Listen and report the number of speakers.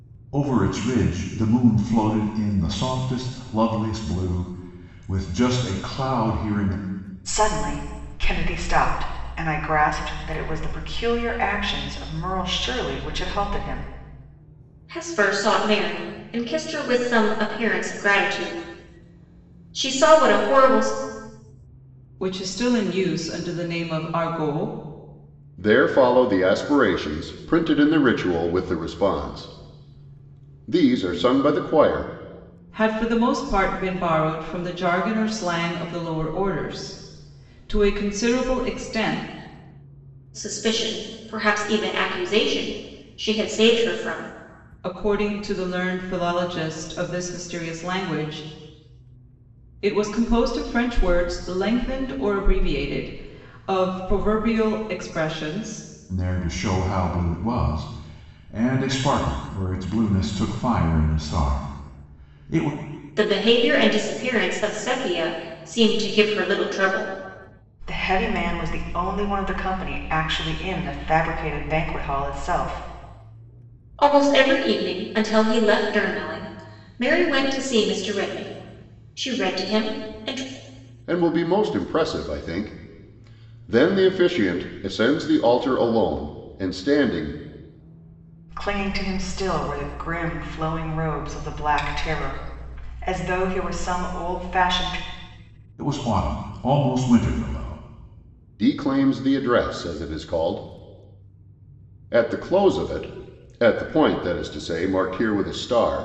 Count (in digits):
5